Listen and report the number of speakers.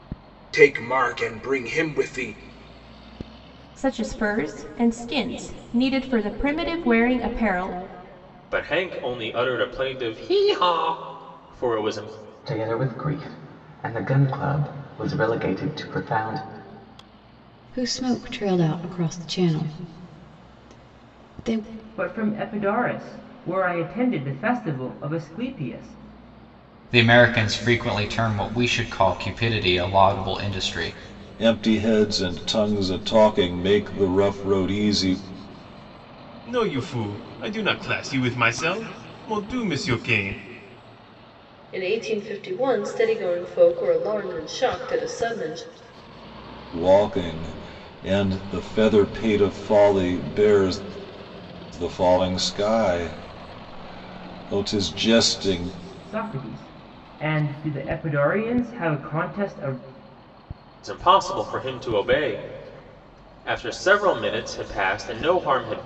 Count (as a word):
ten